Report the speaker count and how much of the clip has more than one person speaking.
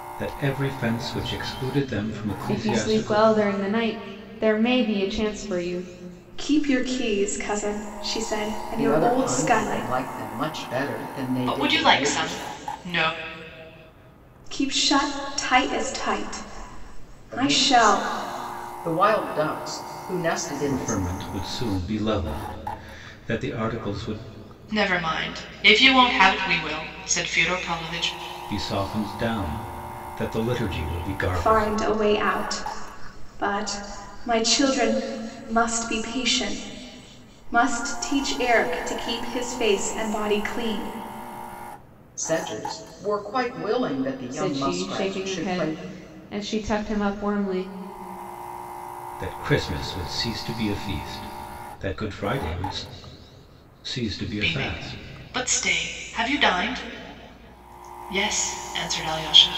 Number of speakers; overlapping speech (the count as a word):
five, about 12%